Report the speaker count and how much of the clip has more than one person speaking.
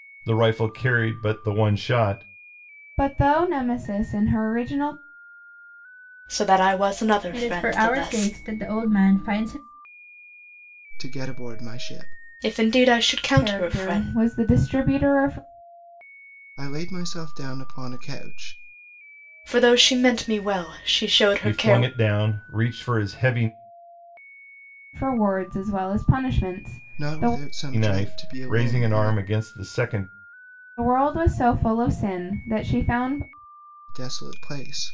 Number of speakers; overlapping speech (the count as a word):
five, about 13%